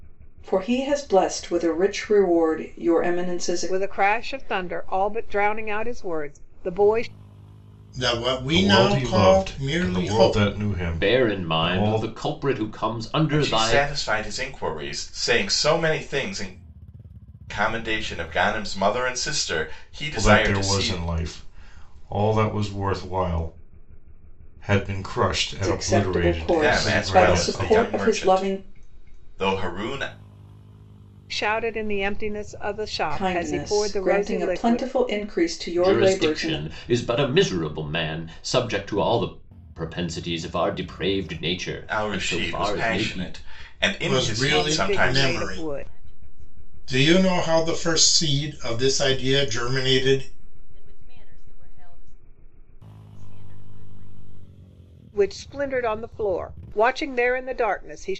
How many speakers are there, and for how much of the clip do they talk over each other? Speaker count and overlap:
7, about 35%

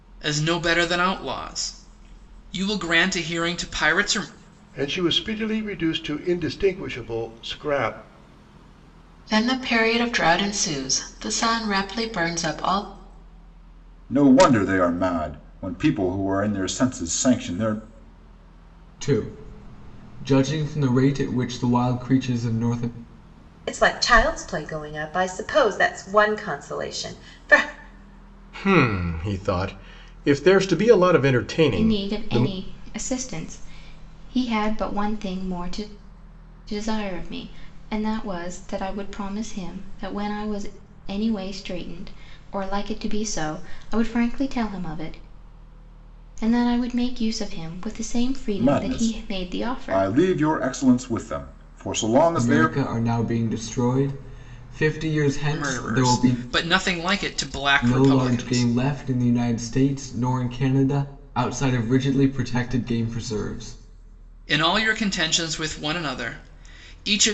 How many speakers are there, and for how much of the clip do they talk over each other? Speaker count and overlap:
8, about 6%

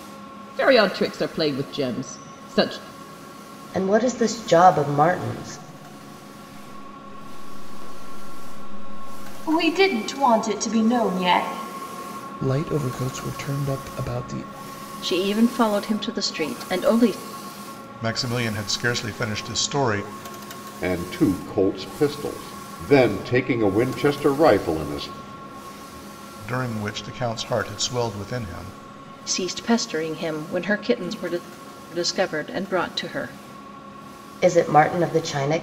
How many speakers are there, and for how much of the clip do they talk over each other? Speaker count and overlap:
8, no overlap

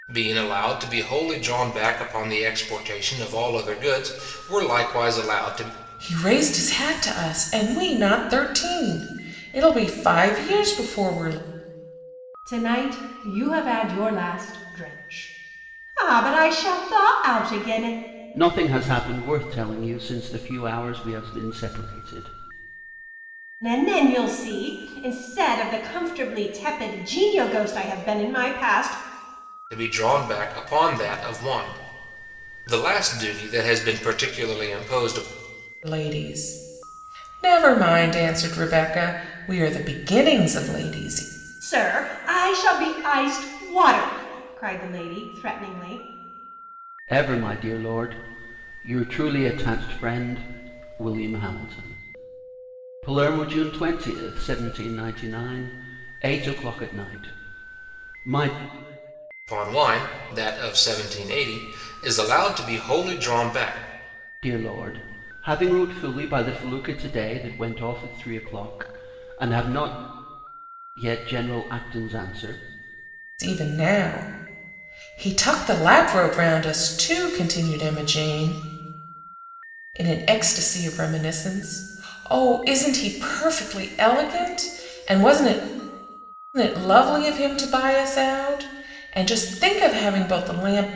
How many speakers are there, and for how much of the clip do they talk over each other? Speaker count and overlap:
4, no overlap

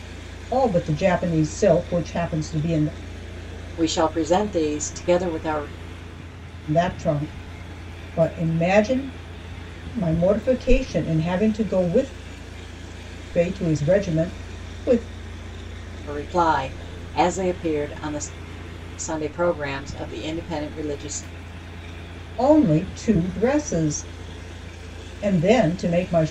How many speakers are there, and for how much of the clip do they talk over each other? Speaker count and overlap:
2, no overlap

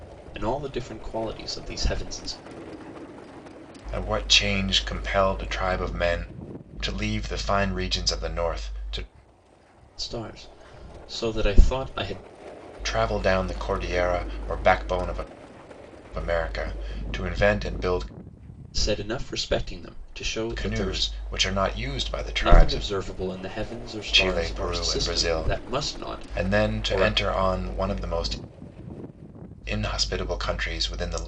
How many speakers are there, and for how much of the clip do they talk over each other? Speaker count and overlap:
2, about 11%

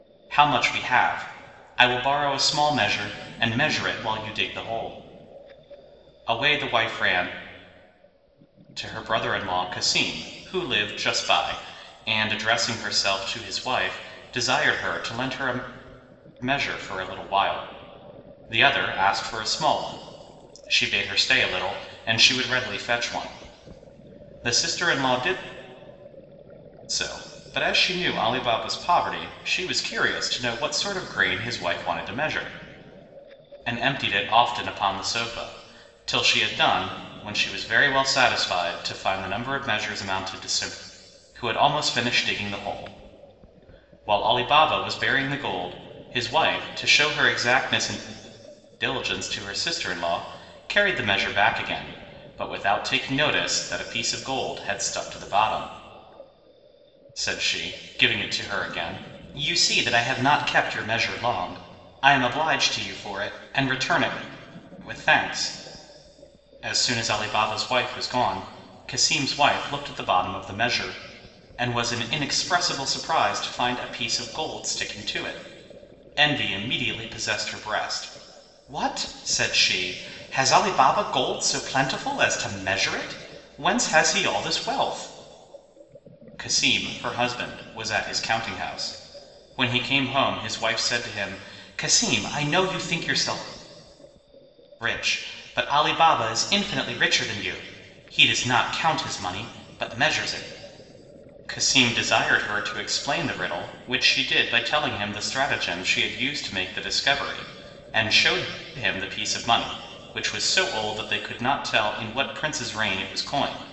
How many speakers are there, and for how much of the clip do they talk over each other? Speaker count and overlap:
1, no overlap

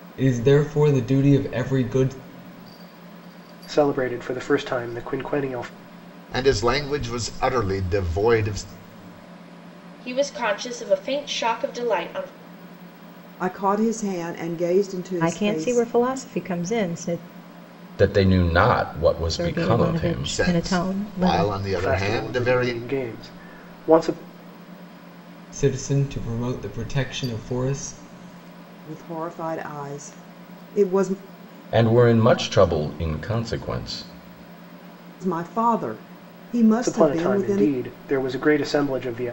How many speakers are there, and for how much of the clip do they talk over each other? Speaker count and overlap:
7, about 12%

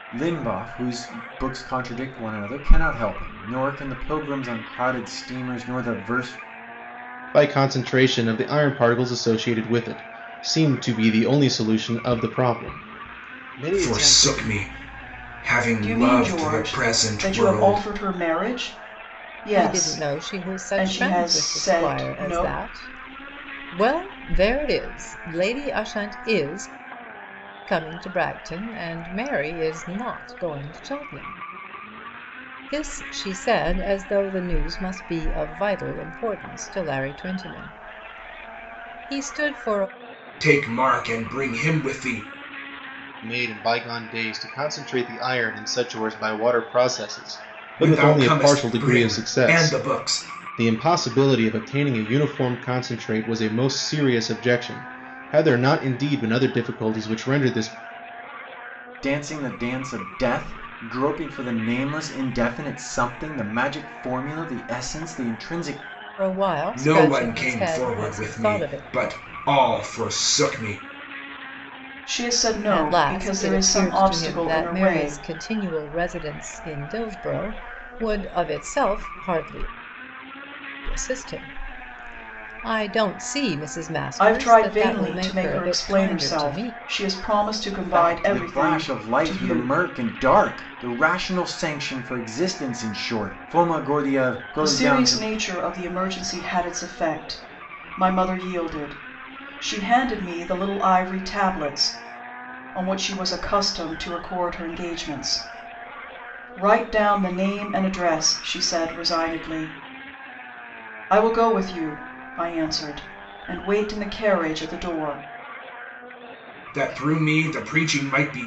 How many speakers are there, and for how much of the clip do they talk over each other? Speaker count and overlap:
5, about 15%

